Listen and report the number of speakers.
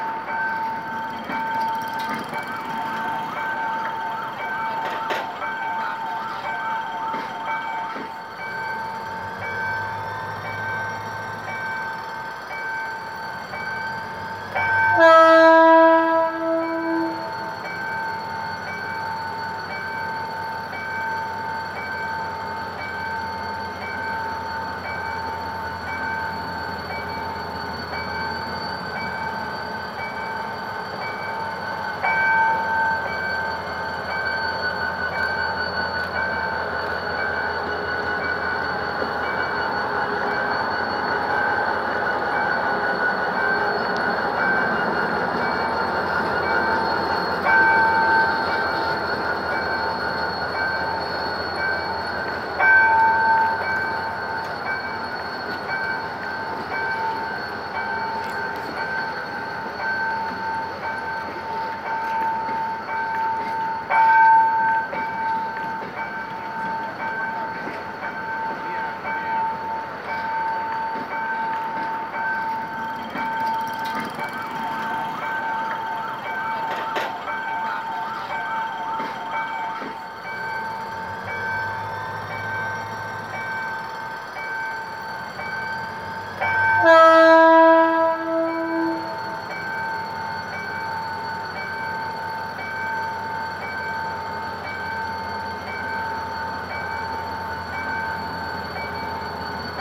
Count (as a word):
zero